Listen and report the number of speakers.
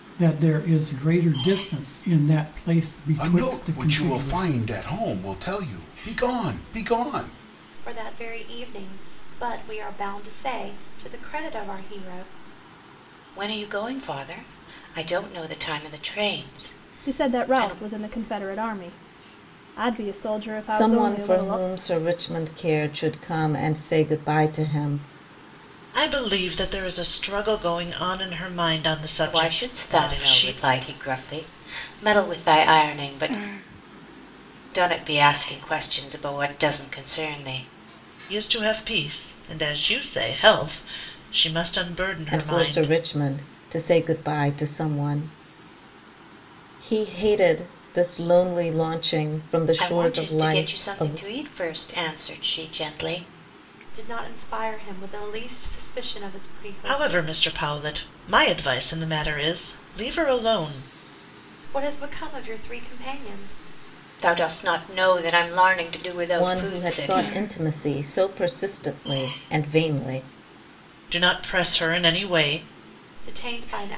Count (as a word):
seven